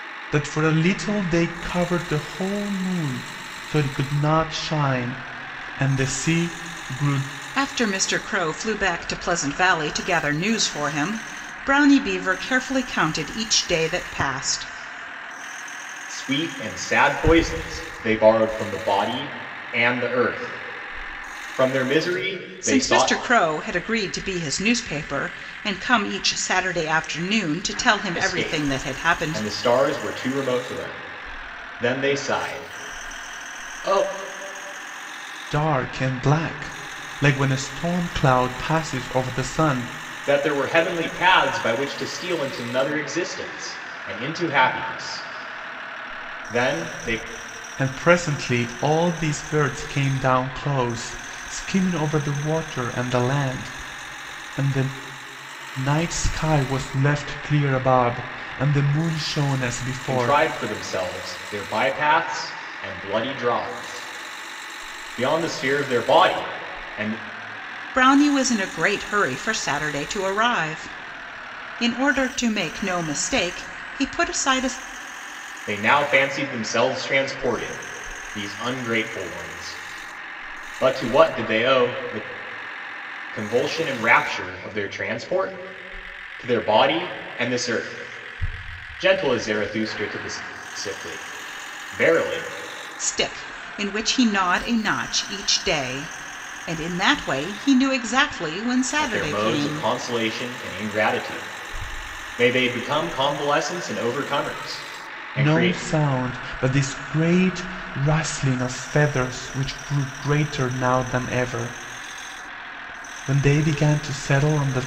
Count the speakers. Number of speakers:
three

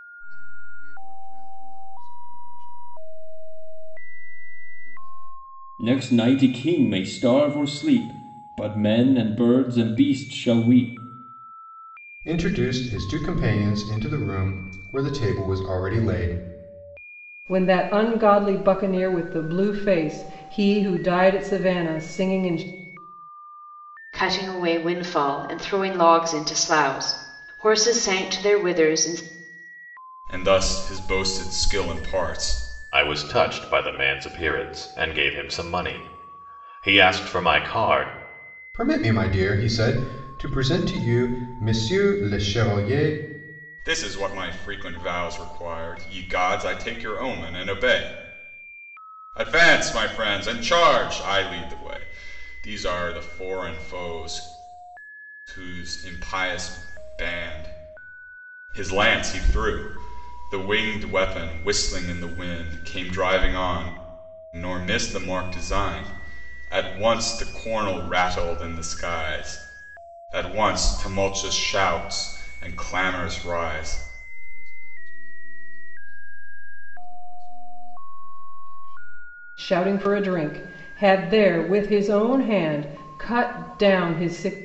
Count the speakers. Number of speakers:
seven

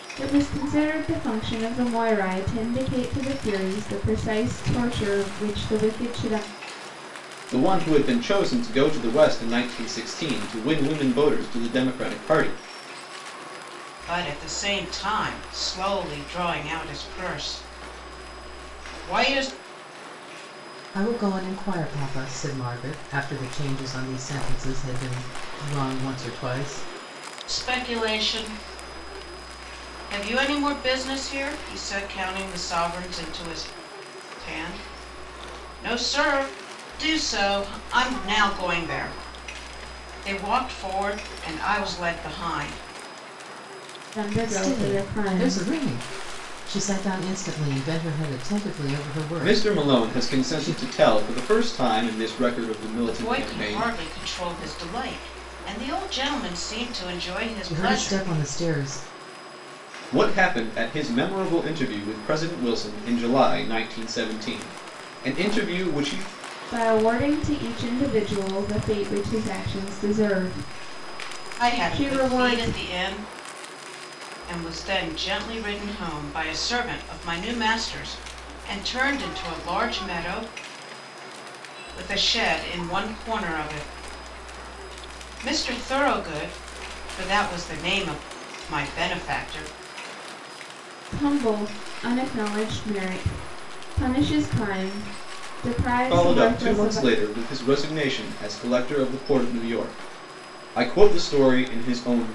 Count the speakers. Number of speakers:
four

